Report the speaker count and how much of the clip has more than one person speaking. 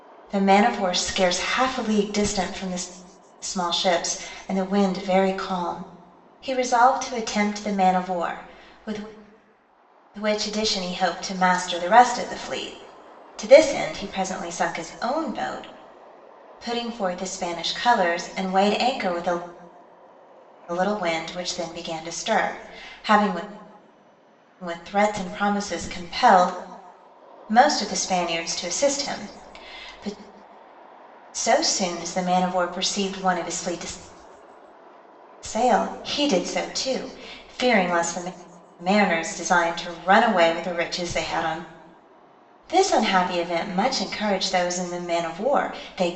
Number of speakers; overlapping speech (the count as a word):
one, no overlap